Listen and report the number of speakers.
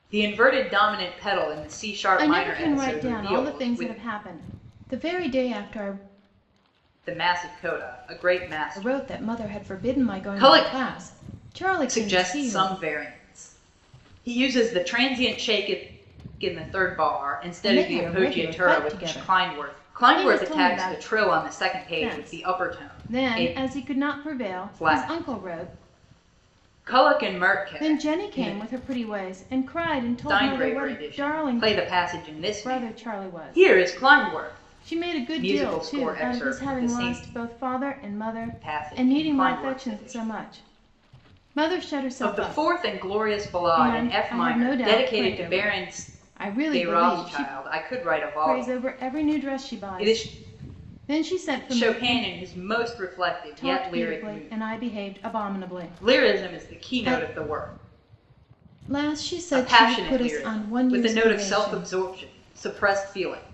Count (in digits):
2